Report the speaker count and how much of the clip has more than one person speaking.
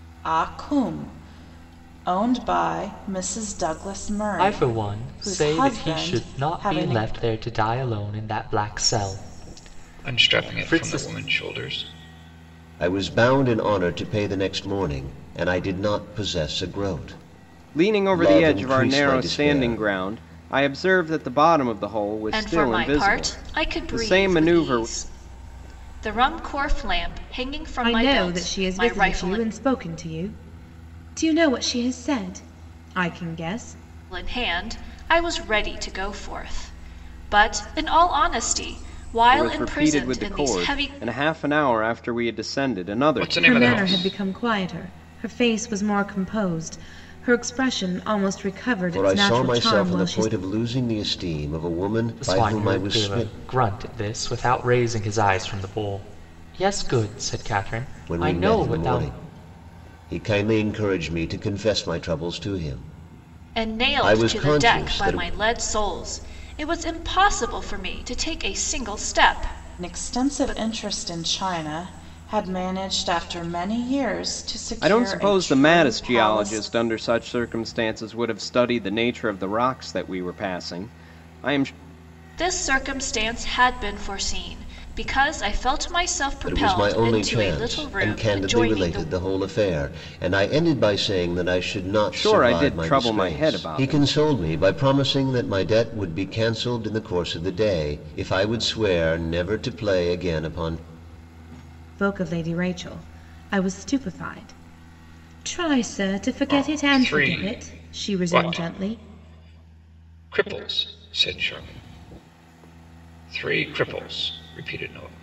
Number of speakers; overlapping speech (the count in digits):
7, about 25%